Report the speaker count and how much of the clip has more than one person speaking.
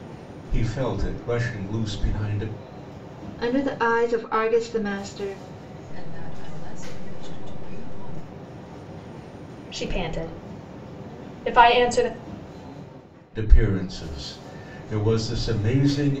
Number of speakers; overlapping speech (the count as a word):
four, no overlap